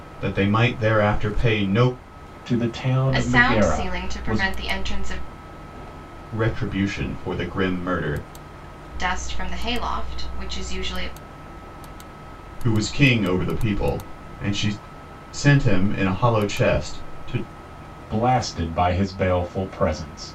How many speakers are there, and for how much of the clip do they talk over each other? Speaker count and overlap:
three, about 7%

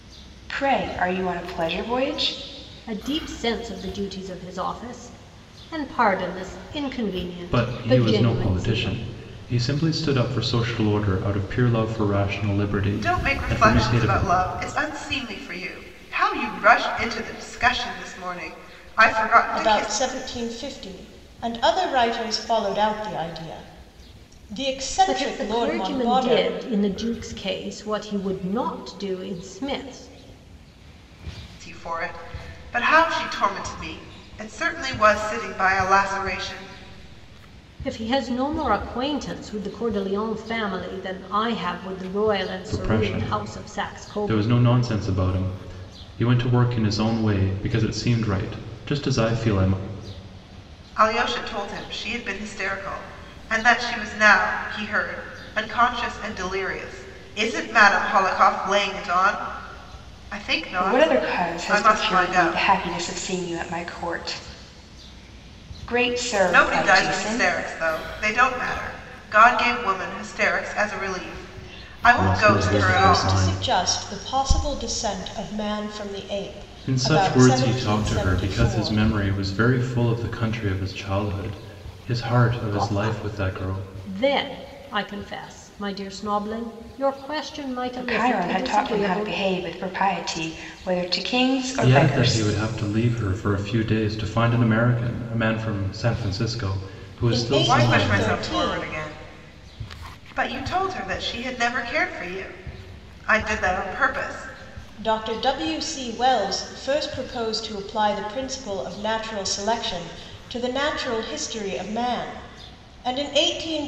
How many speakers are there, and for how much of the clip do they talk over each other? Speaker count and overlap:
five, about 16%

